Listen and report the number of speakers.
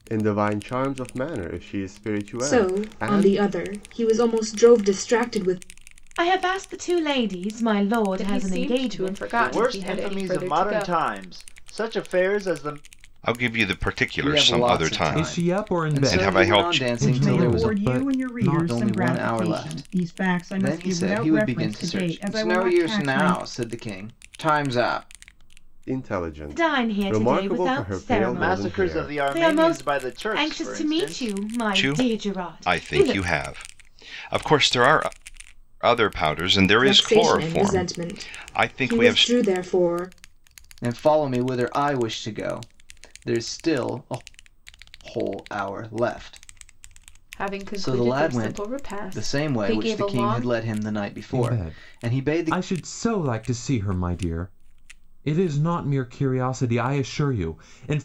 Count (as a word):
nine